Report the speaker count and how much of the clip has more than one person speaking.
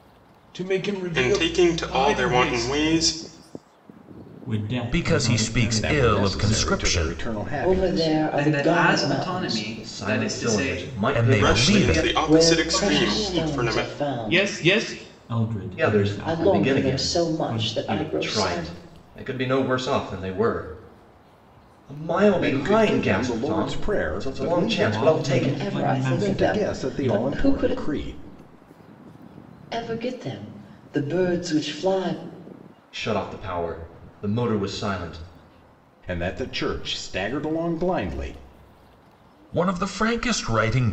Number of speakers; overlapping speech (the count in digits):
8, about 46%